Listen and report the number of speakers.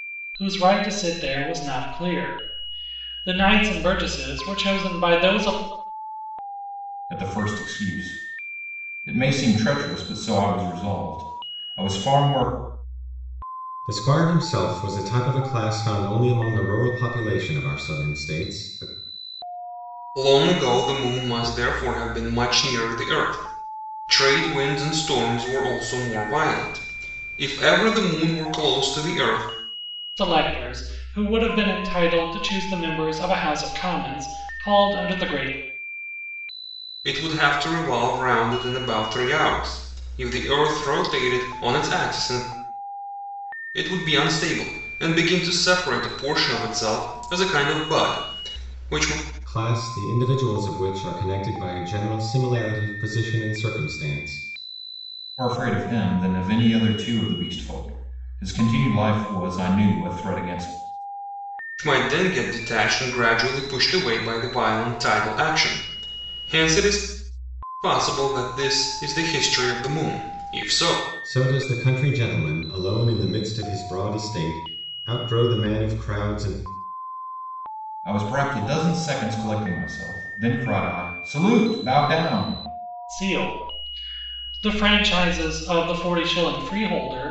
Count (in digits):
4